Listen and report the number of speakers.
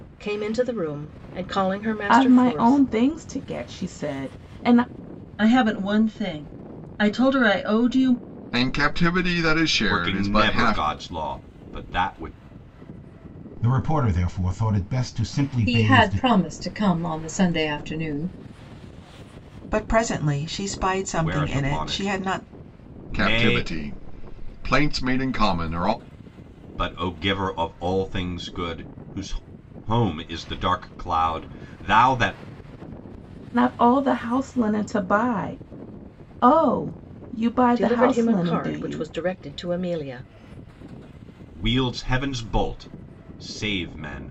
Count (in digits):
8